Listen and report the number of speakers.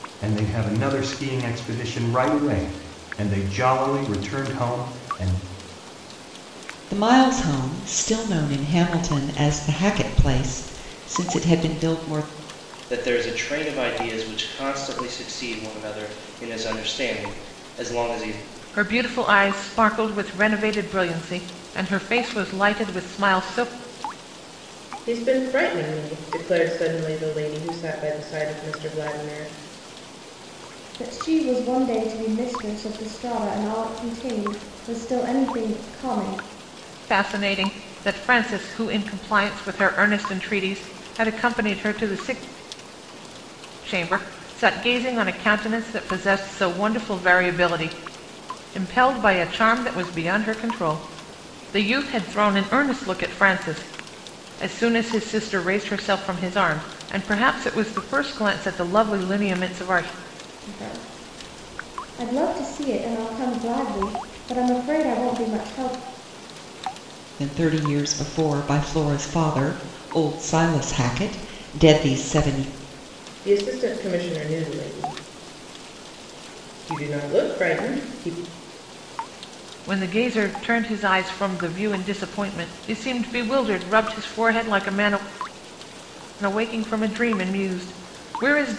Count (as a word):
six